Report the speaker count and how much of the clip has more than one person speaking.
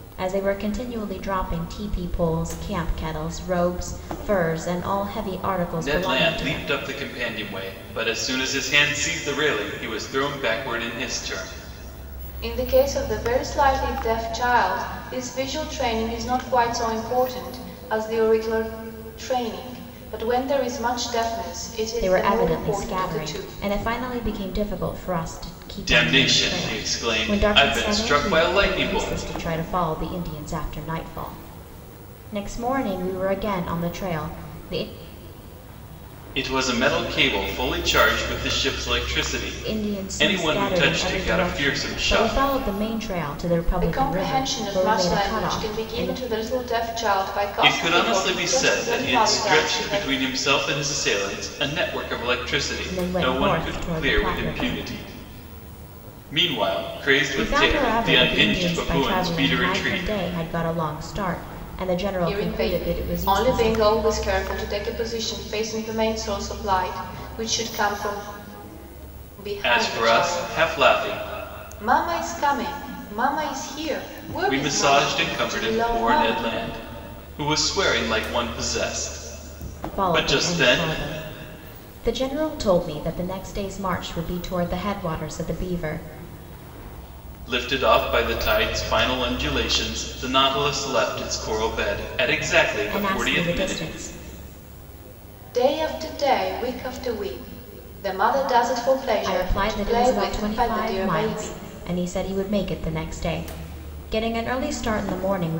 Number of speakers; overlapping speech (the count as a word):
three, about 26%